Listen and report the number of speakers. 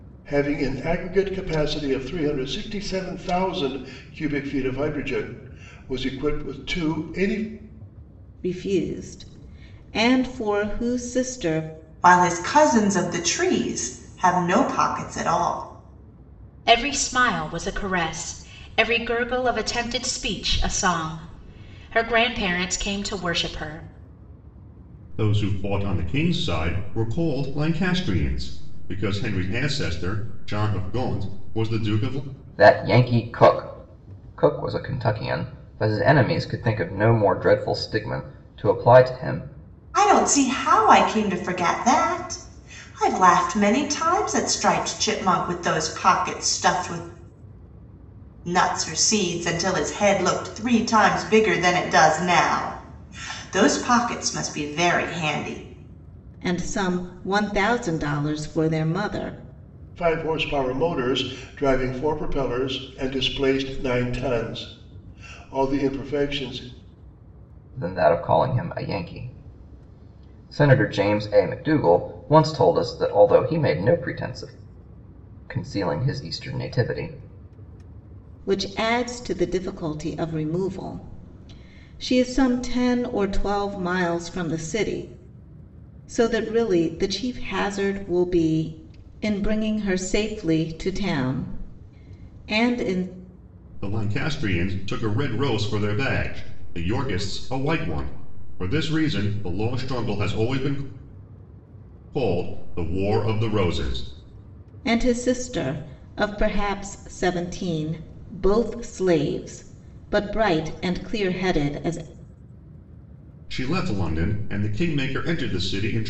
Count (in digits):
6